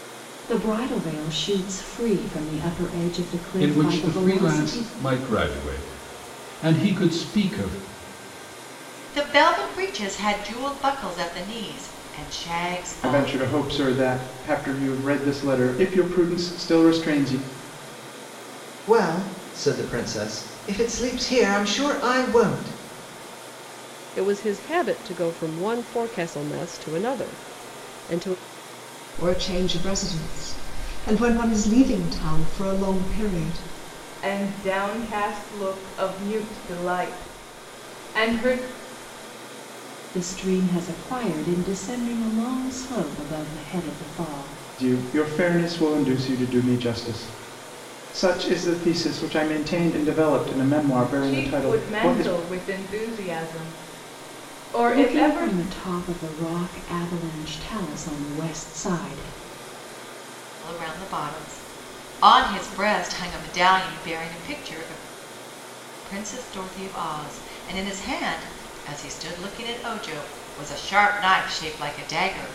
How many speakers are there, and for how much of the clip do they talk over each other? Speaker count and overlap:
8, about 5%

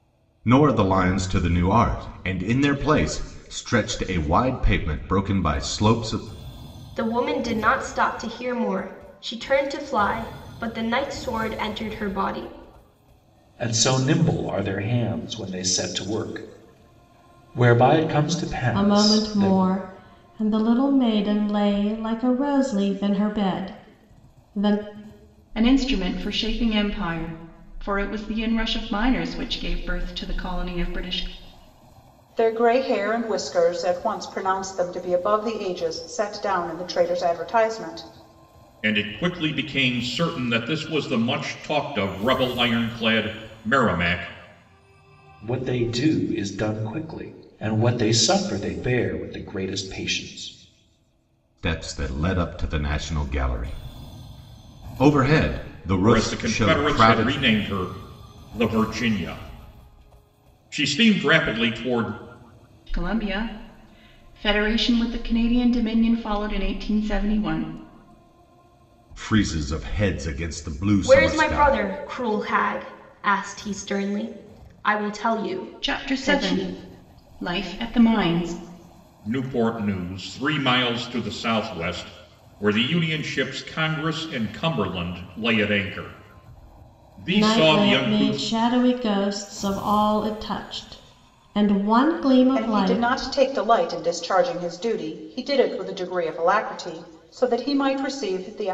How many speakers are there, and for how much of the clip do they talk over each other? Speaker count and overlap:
7, about 6%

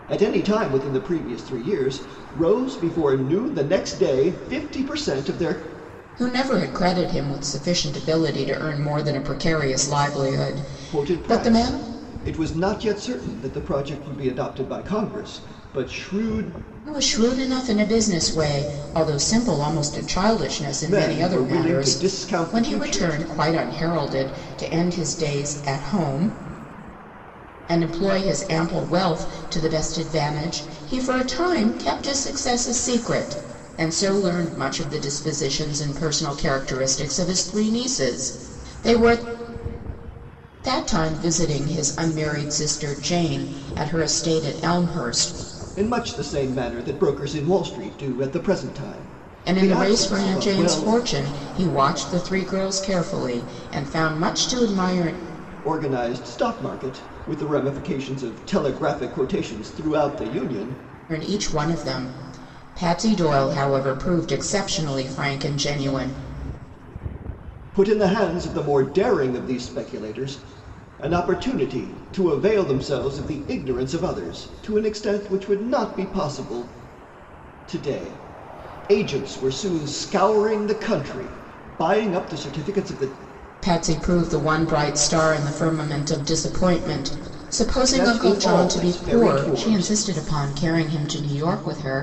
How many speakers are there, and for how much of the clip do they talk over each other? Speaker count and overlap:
2, about 7%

